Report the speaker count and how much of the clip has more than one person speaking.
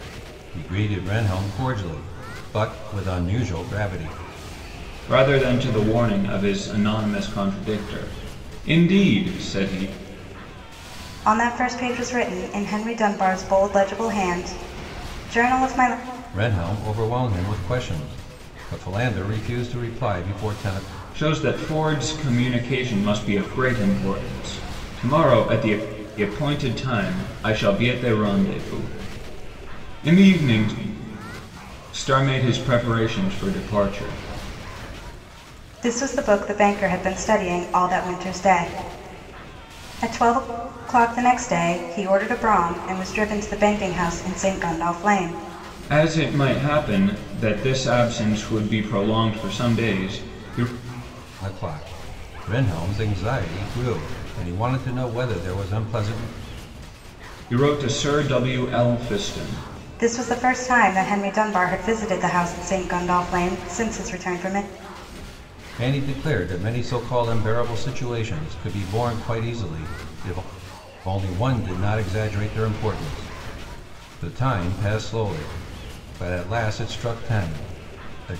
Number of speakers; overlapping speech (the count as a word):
three, no overlap